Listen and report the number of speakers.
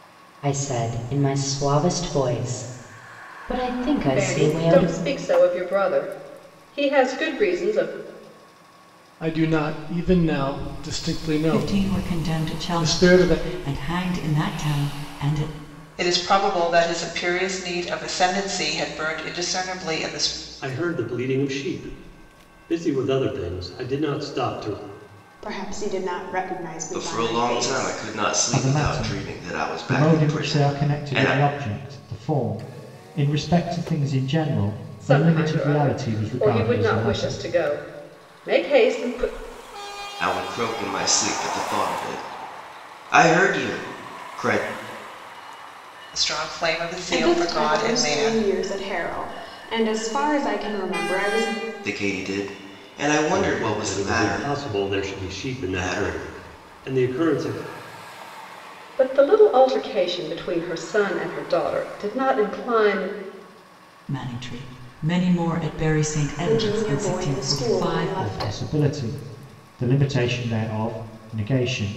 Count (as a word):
nine